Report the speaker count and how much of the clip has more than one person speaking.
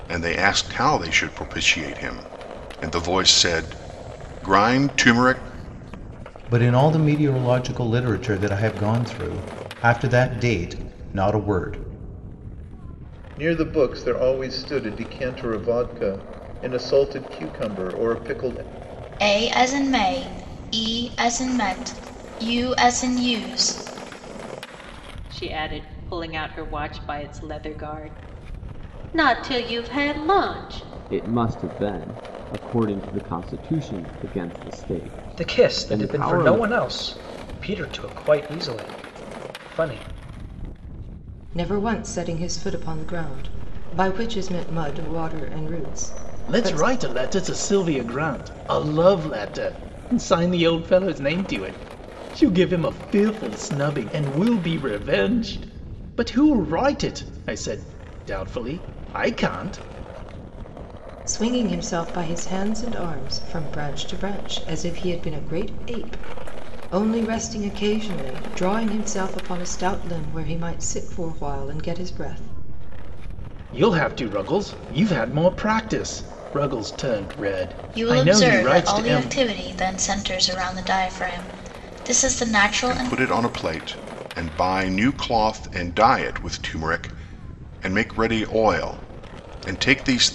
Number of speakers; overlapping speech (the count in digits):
9, about 4%